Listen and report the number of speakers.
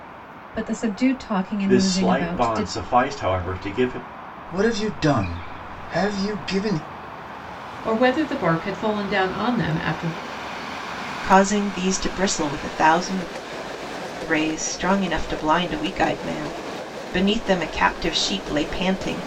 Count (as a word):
five